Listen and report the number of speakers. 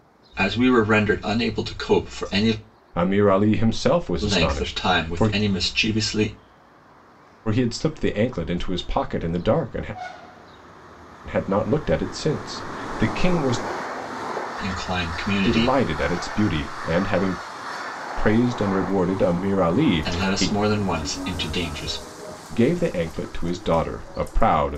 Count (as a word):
two